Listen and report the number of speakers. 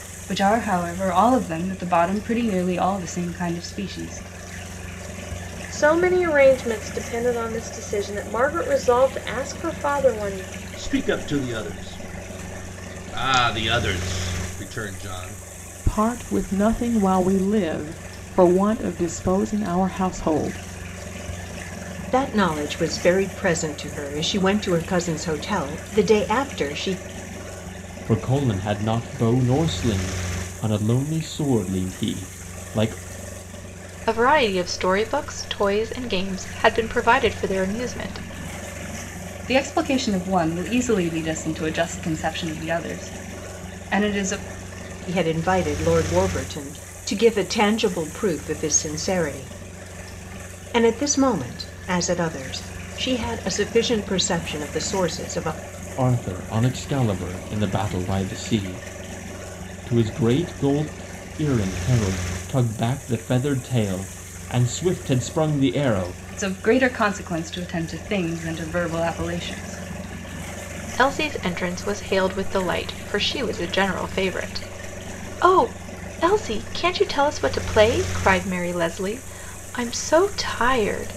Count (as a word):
seven